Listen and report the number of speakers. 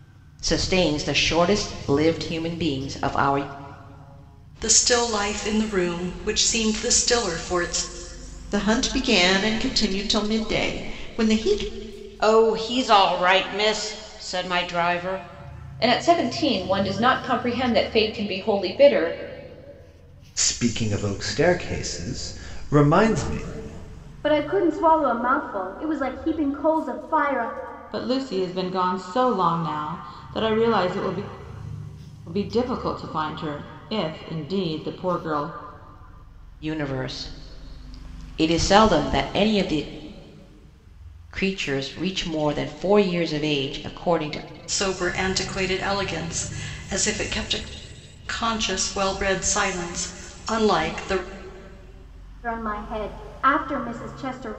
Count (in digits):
8